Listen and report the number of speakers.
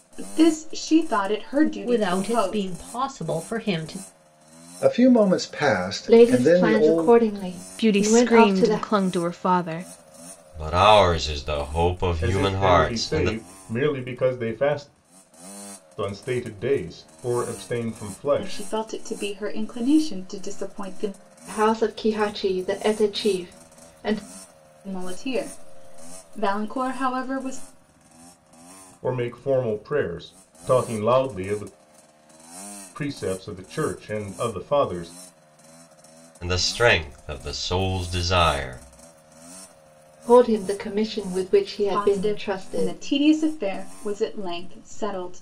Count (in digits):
7